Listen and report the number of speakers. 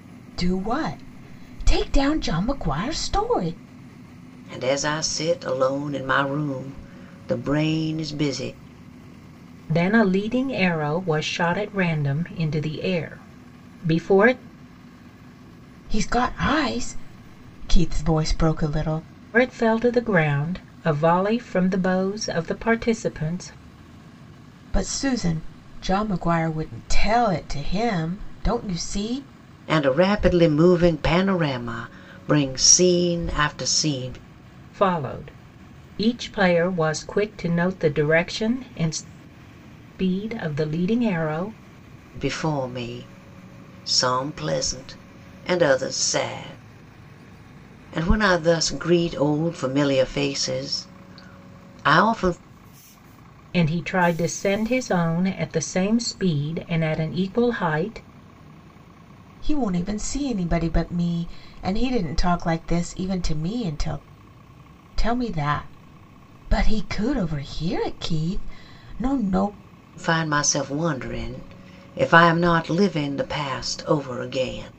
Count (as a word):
three